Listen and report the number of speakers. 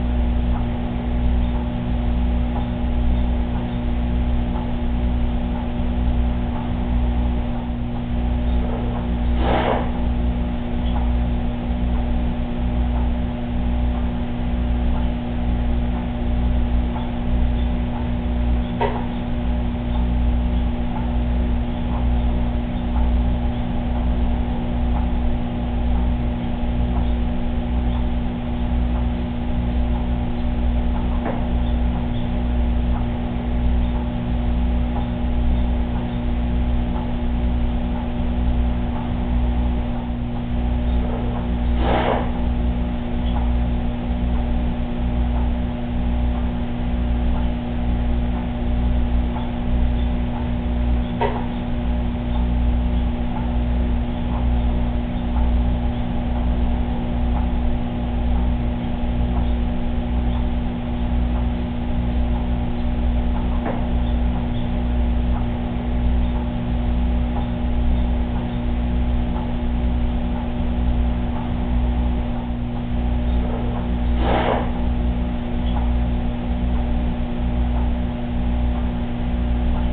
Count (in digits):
0